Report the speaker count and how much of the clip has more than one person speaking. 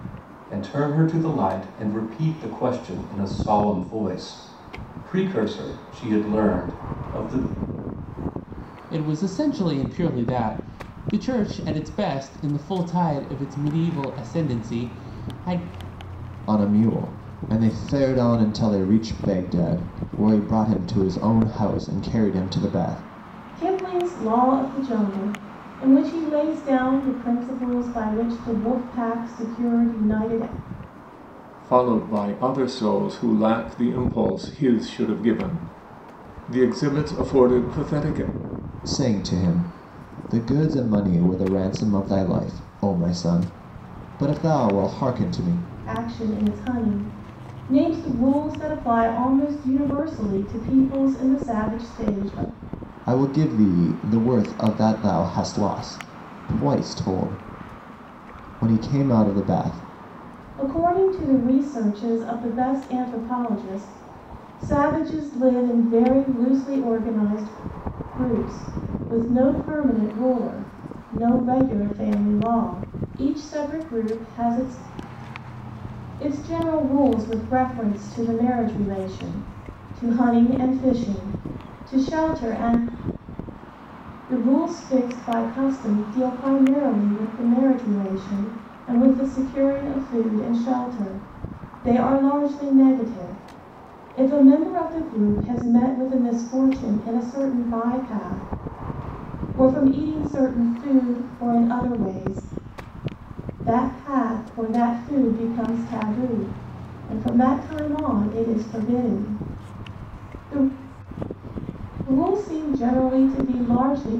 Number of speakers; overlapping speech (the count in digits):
5, no overlap